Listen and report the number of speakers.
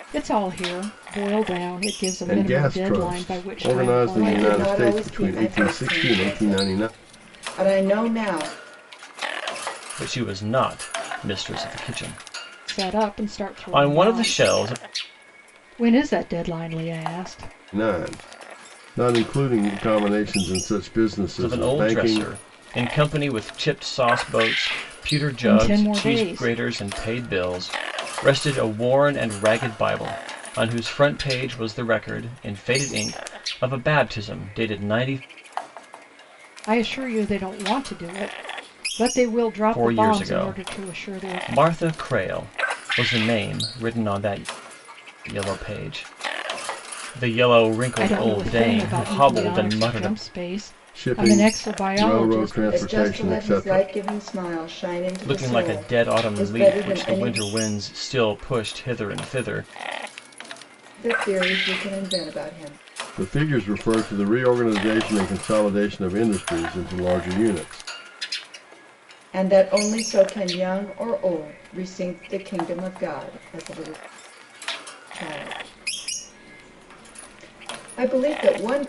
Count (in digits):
4